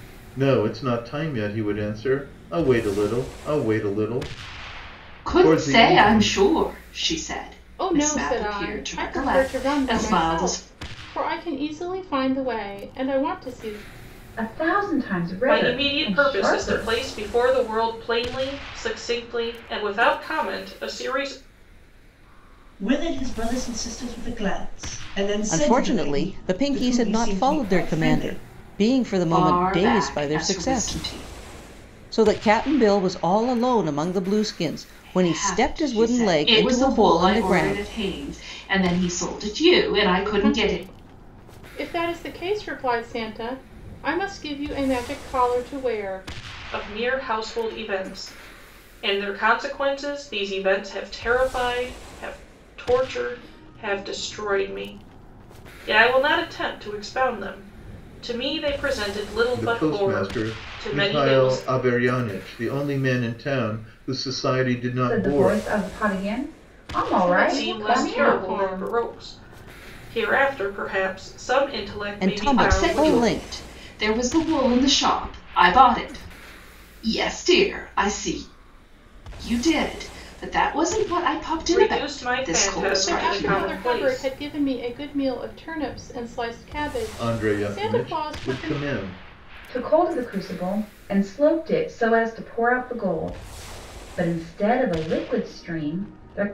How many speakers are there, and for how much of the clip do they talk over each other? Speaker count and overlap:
7, about 25%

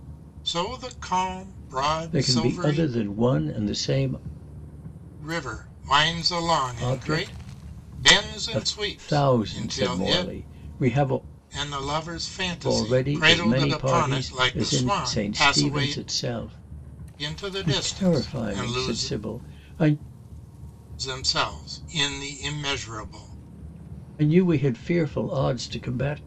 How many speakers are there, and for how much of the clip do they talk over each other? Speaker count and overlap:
2, about 32%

